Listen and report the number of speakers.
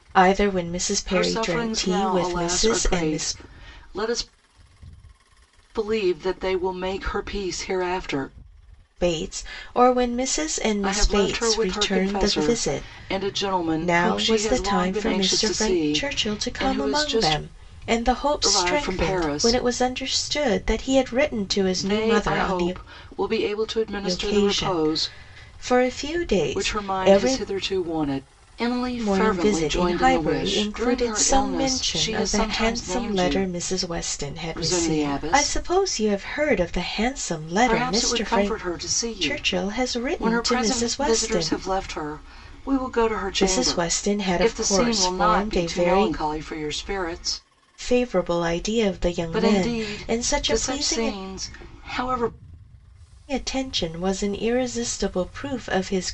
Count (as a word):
two